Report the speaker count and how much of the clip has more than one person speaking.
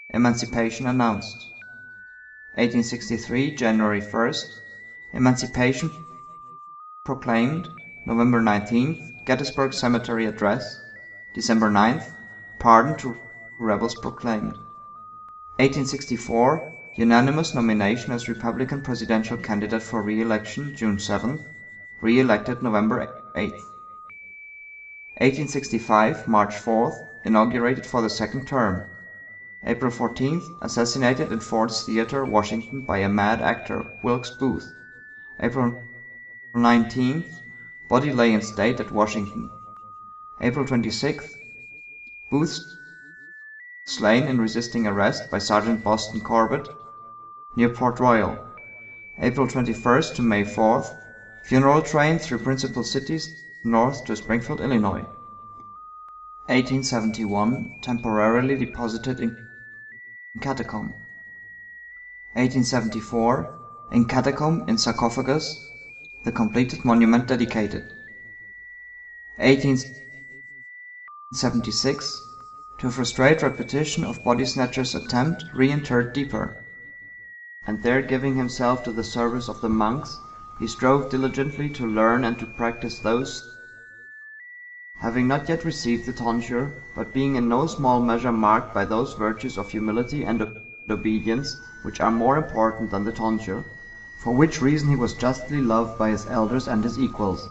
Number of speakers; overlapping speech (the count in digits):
1, no overlap